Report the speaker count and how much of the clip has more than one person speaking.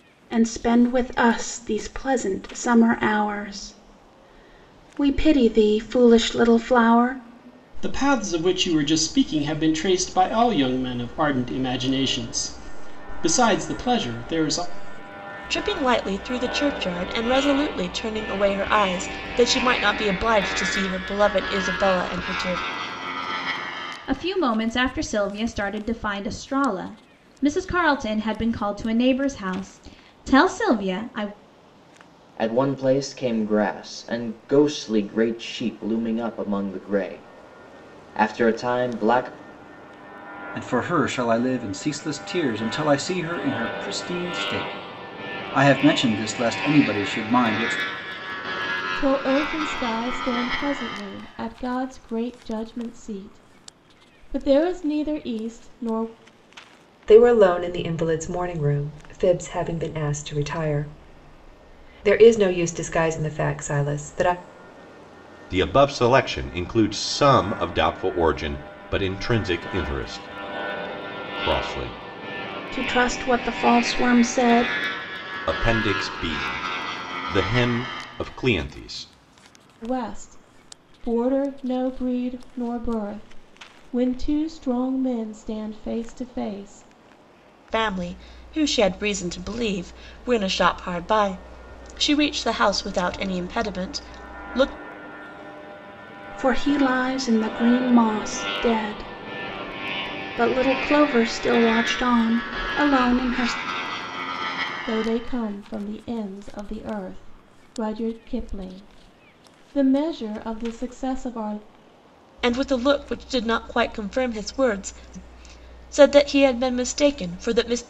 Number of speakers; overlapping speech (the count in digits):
9, no overlap